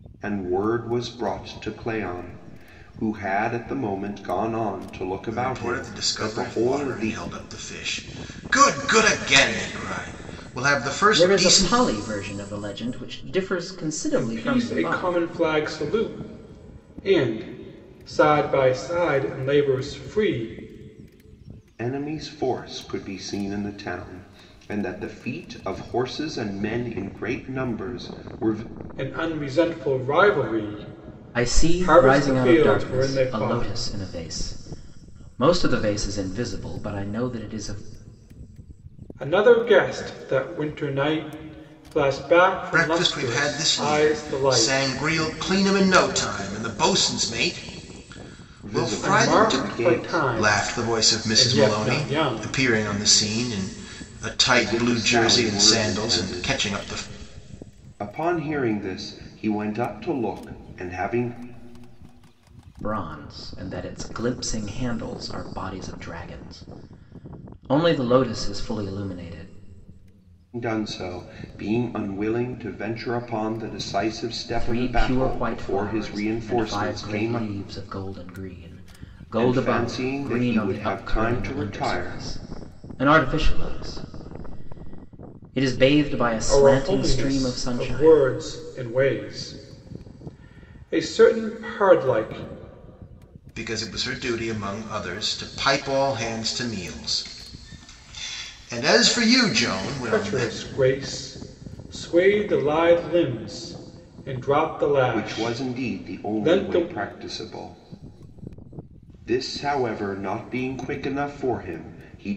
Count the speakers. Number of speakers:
four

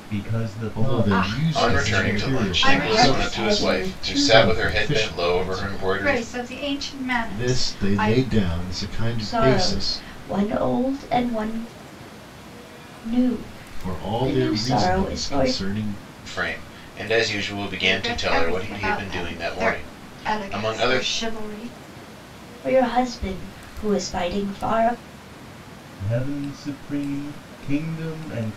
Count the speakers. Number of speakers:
five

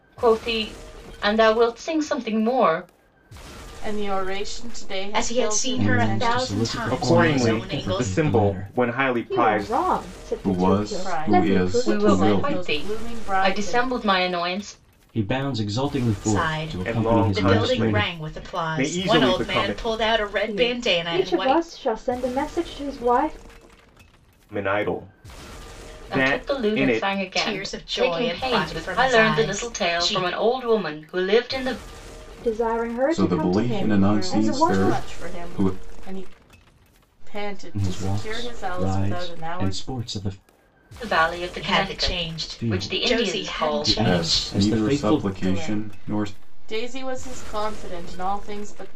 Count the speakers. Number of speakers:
seven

